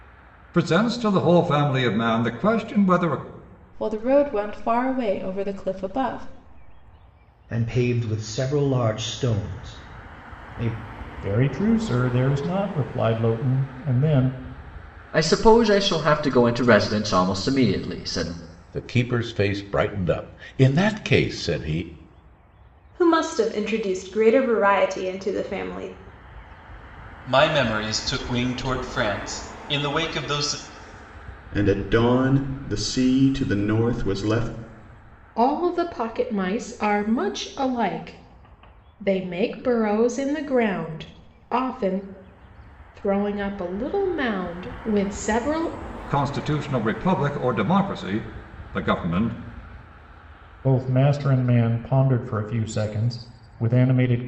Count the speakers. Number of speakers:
10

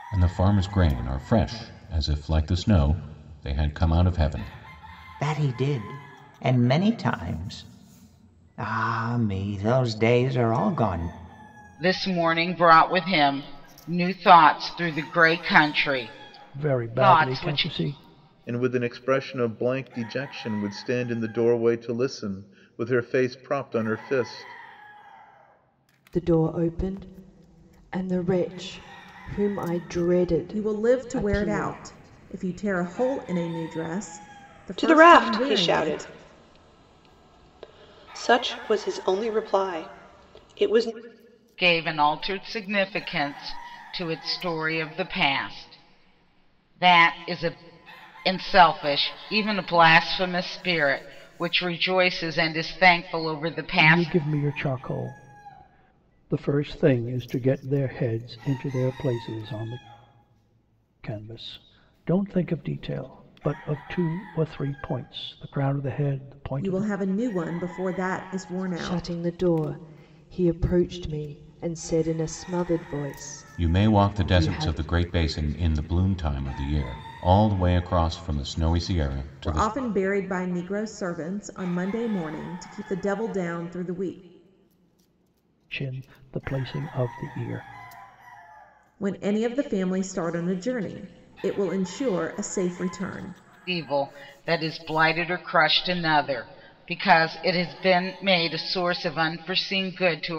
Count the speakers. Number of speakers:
8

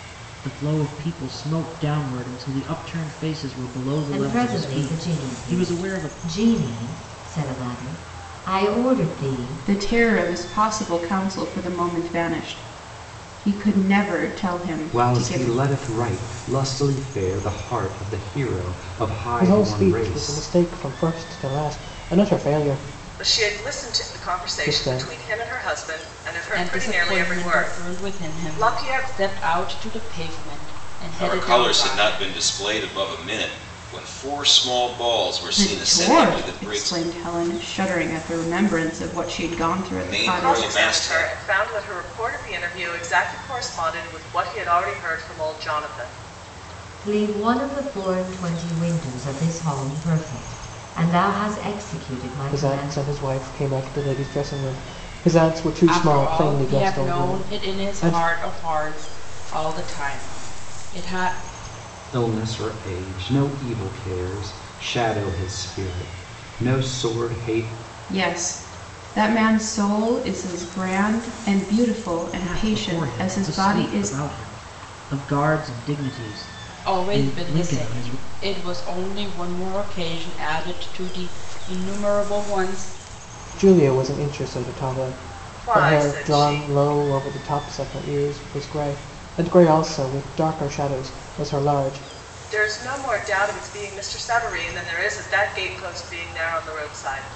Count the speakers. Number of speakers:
8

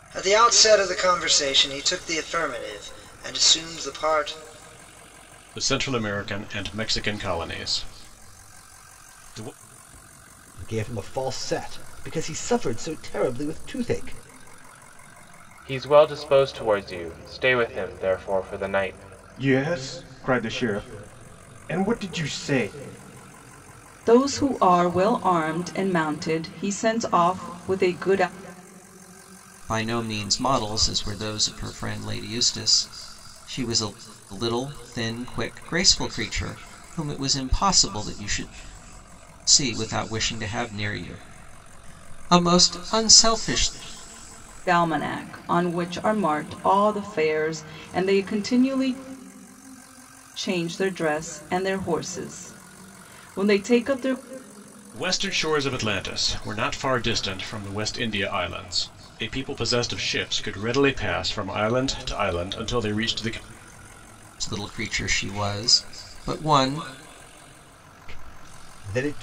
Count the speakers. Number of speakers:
7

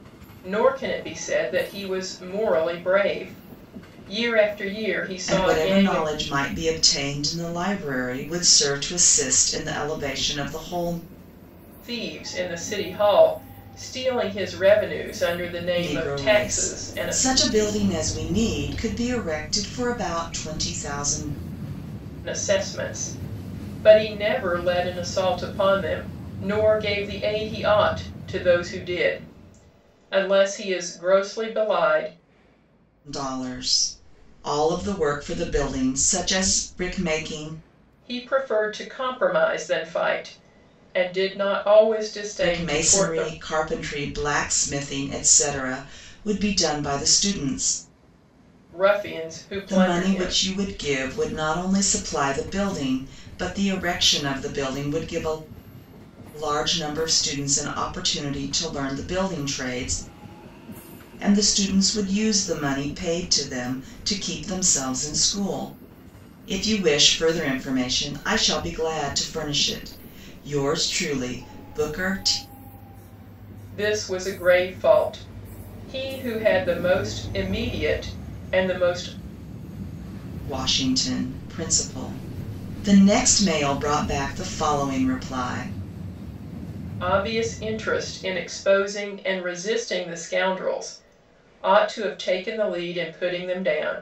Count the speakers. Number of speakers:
2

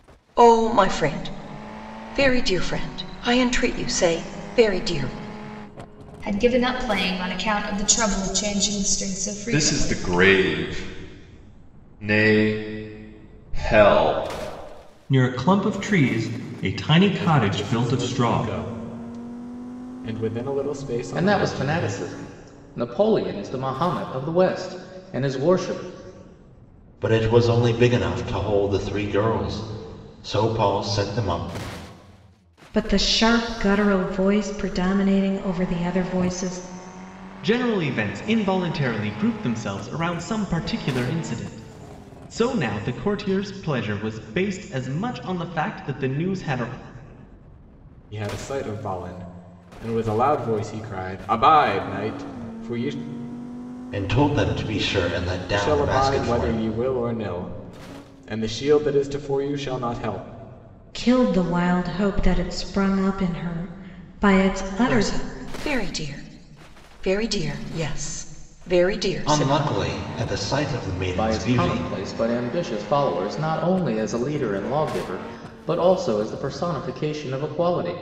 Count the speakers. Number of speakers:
9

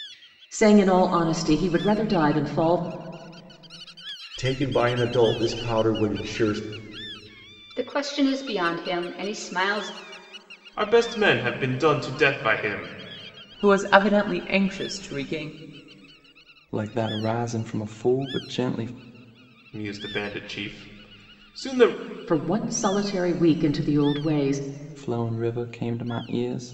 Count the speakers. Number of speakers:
6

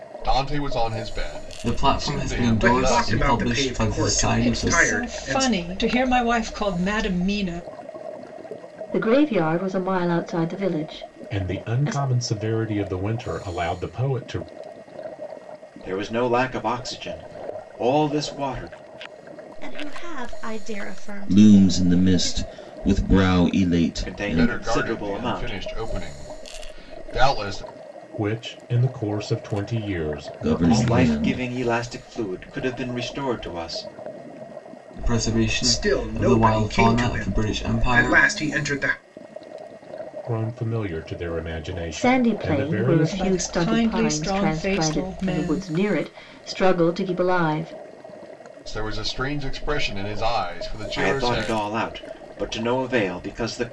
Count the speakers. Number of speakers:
9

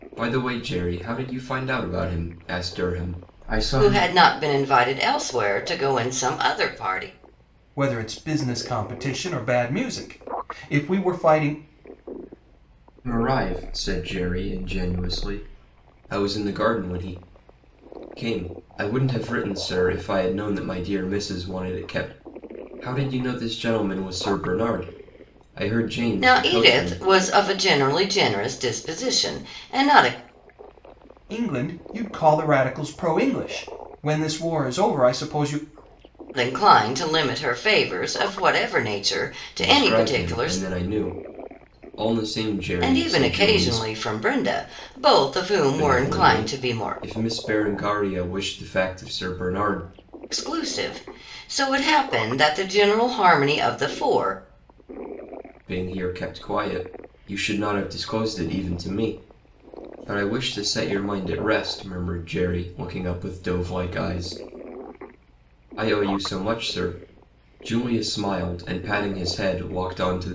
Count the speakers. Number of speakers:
3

